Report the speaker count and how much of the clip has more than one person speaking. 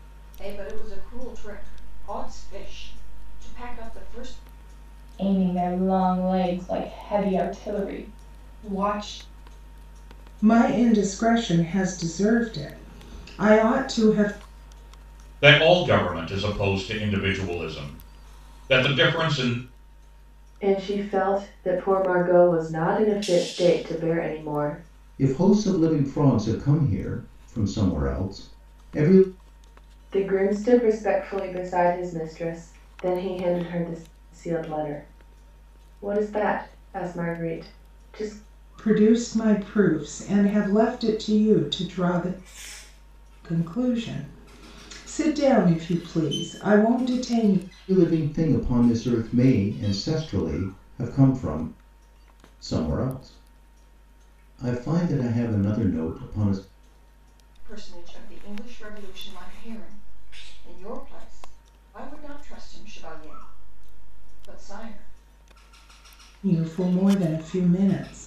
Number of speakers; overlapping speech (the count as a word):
six, no overlap